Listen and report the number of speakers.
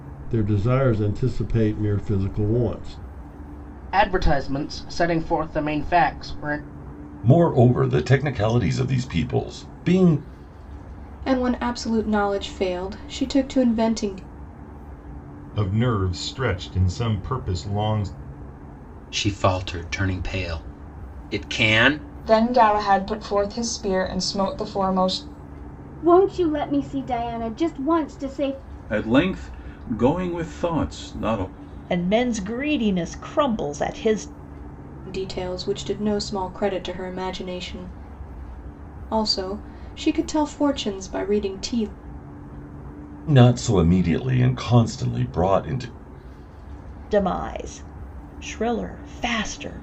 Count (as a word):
ten